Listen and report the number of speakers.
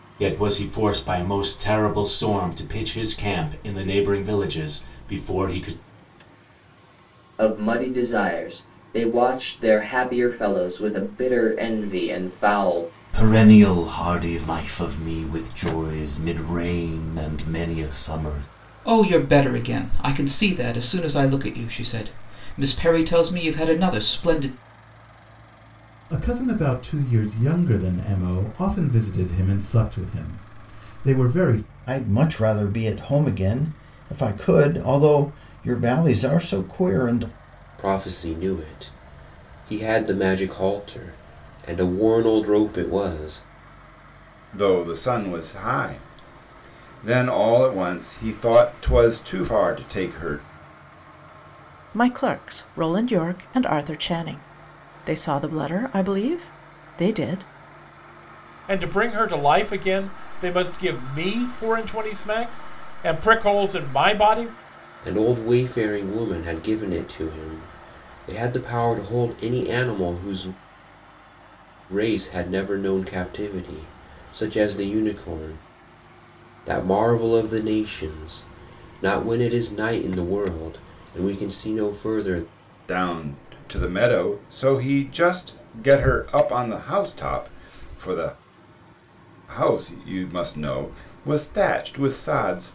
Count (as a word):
ten